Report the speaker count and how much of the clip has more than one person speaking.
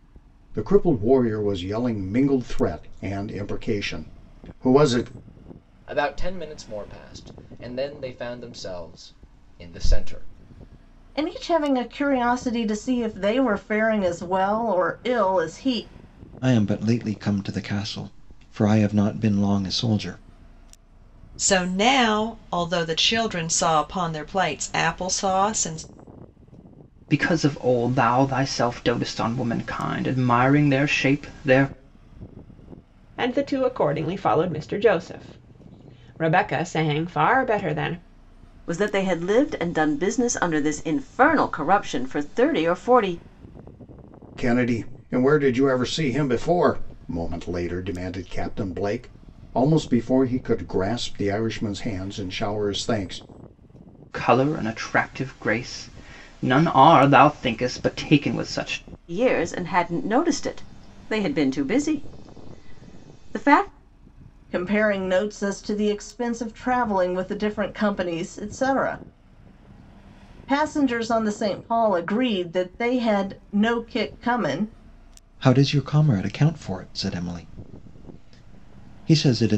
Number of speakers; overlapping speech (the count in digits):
8, no overlap